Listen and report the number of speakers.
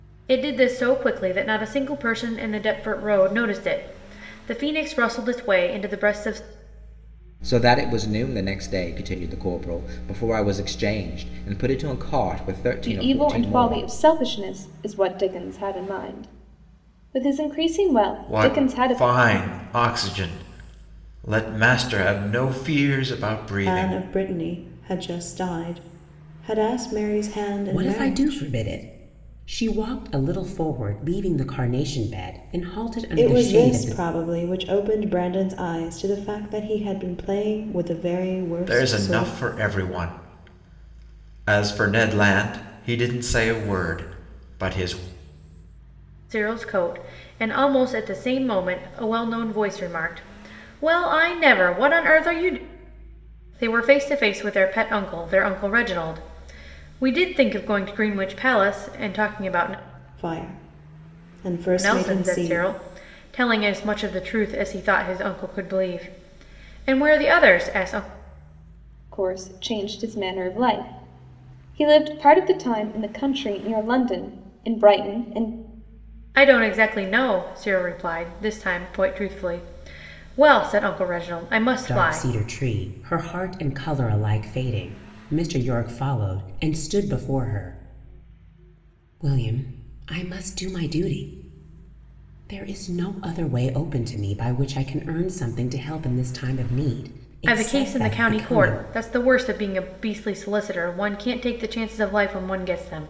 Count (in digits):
6